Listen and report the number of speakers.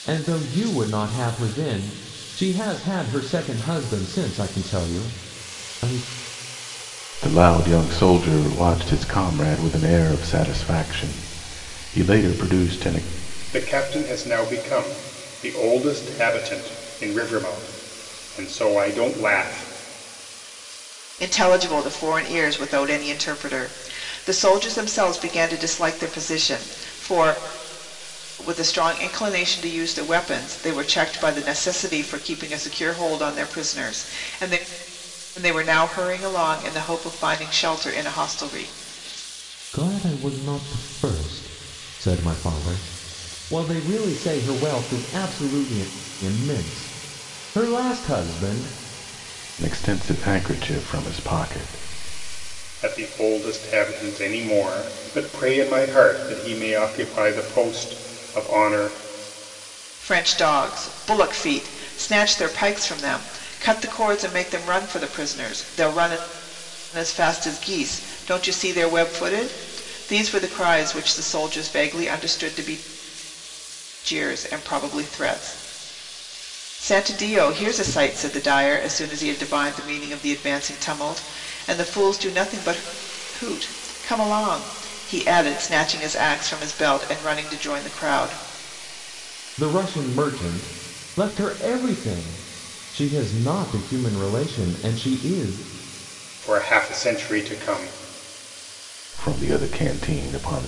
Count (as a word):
four